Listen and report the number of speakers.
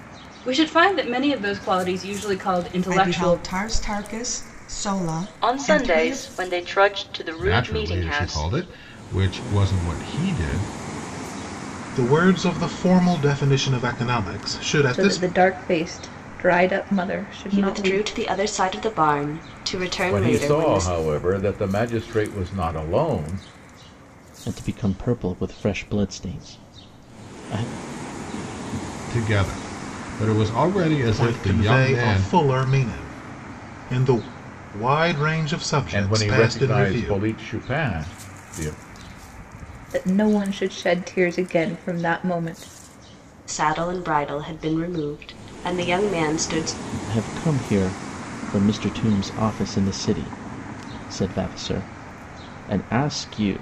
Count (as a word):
nine